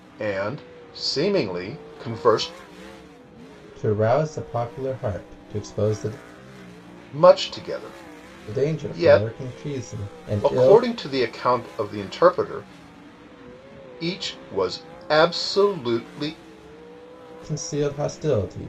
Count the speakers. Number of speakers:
two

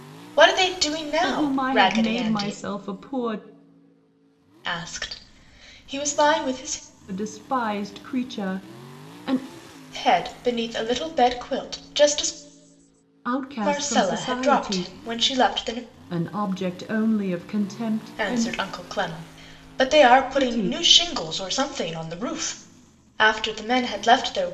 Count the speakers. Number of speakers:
two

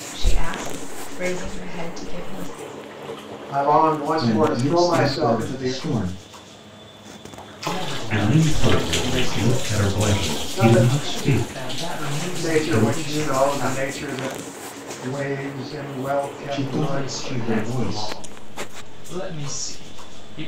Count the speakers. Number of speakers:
five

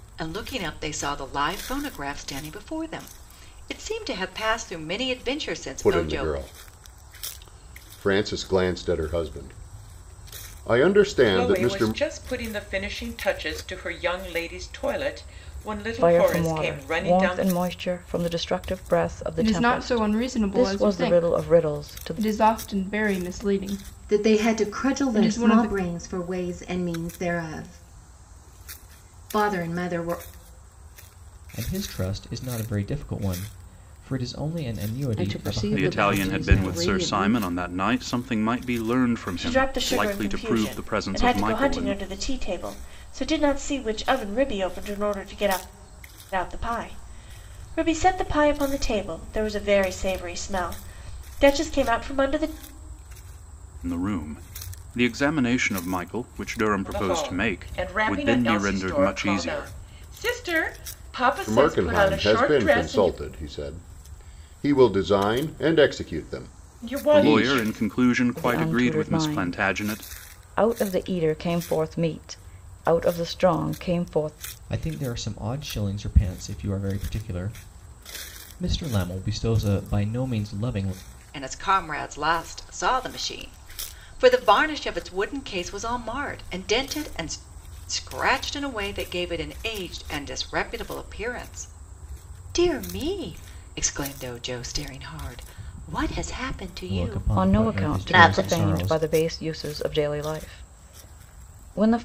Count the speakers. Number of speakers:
ten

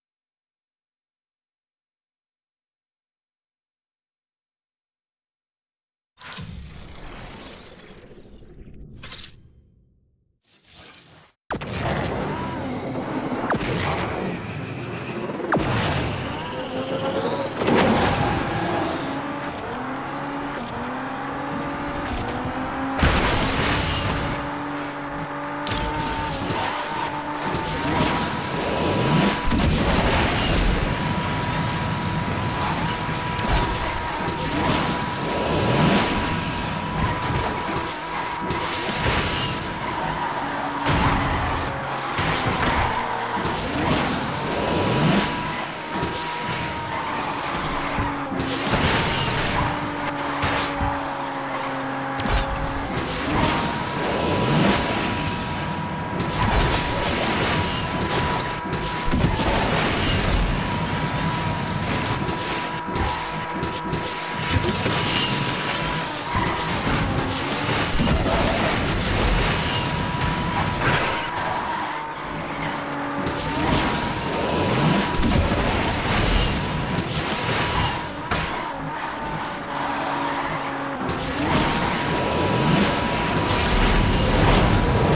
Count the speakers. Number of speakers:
zero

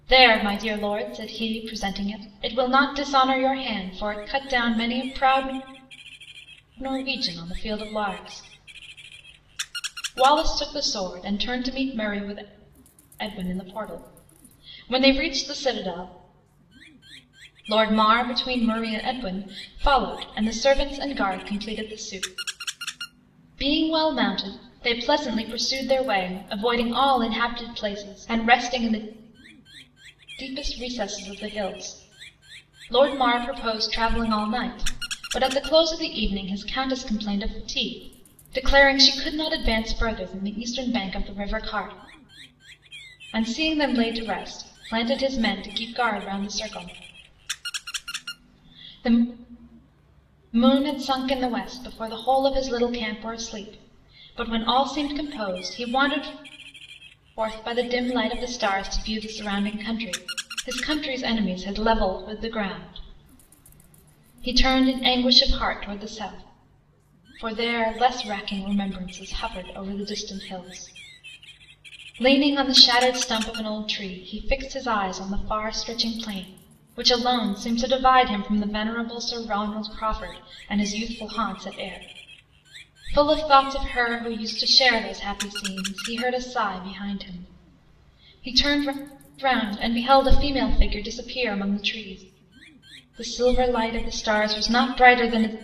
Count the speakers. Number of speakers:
one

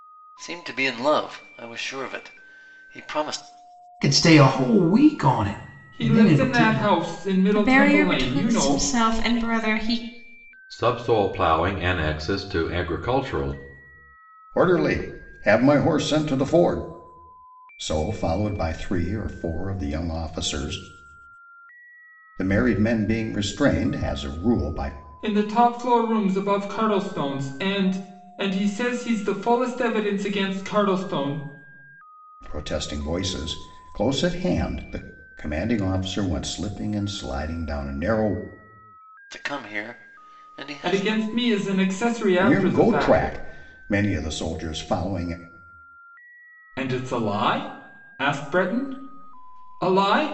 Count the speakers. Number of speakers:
six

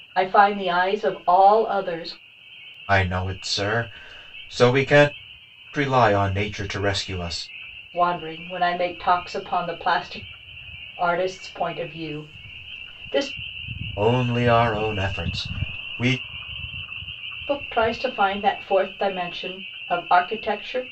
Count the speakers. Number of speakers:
two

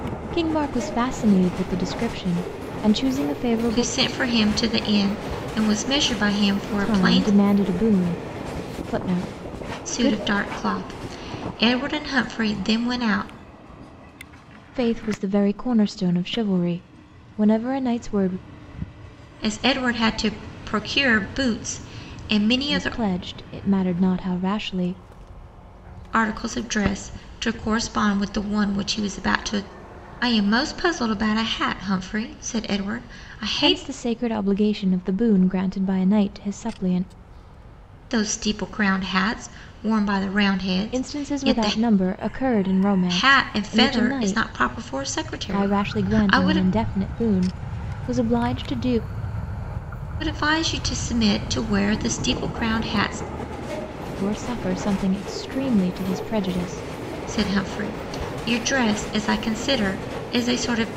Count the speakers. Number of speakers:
two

